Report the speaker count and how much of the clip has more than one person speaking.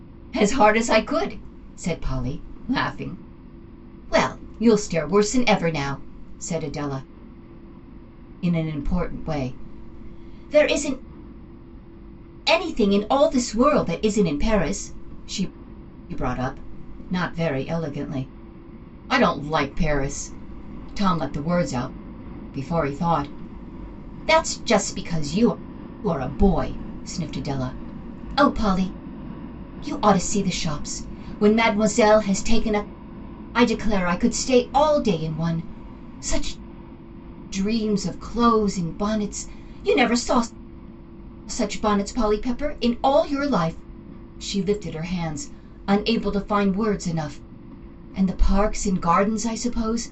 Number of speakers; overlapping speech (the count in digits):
1, no overlap